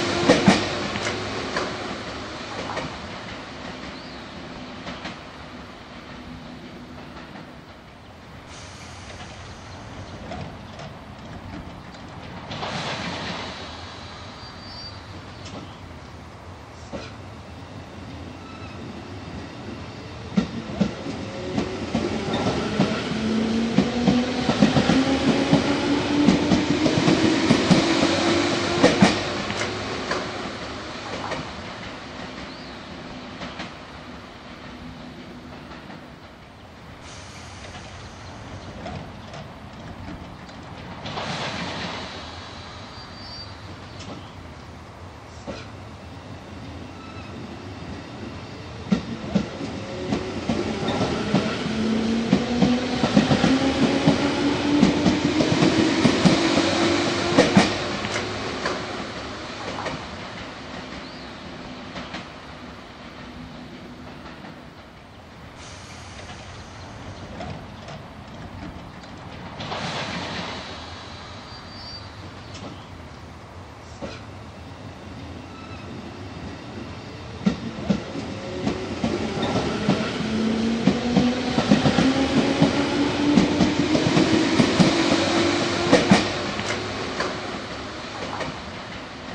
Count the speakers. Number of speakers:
zero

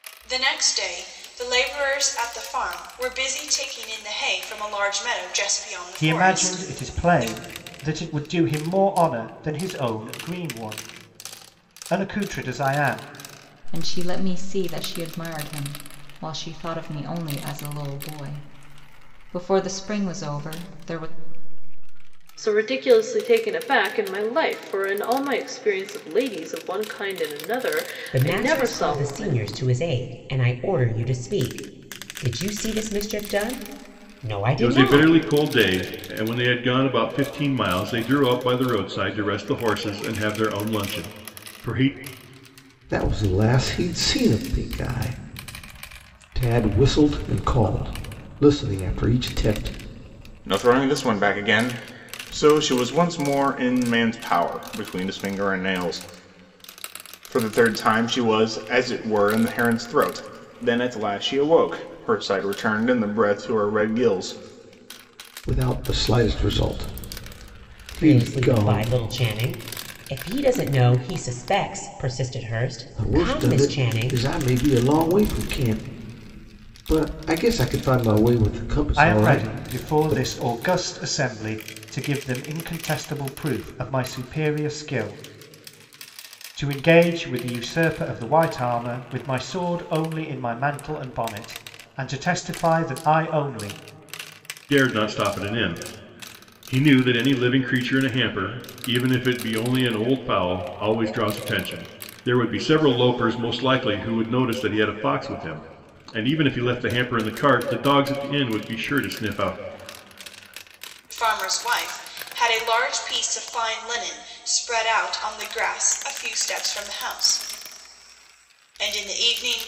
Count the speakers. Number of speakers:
eight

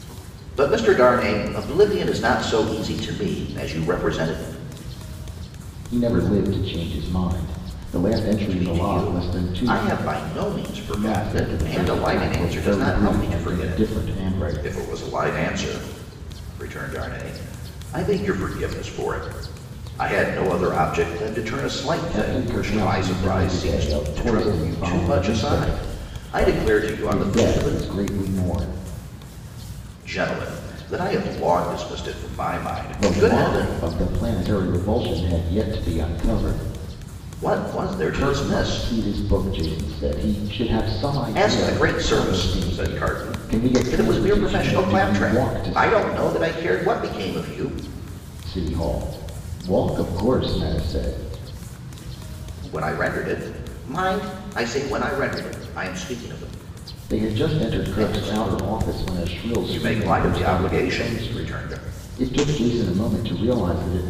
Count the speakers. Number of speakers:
two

